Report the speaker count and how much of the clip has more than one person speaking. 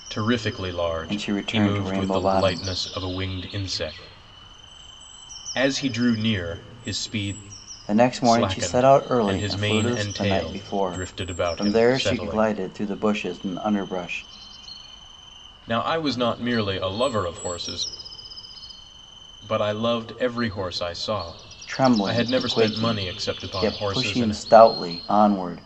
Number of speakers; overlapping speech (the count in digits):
2, about 31%